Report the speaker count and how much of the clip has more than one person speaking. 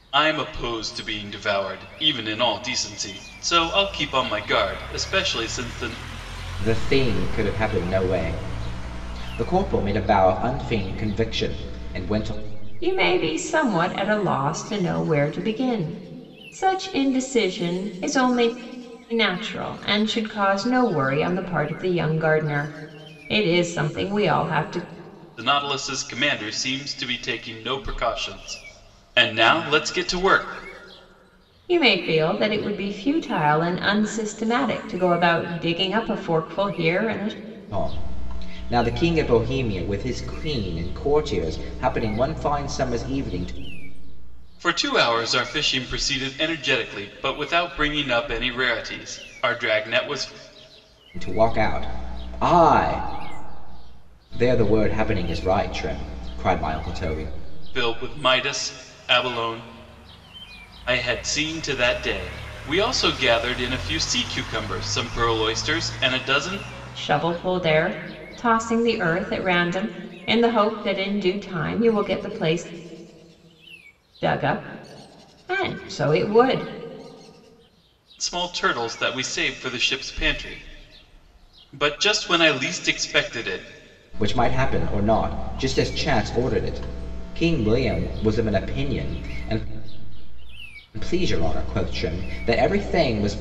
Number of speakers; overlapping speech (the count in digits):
3, no overlap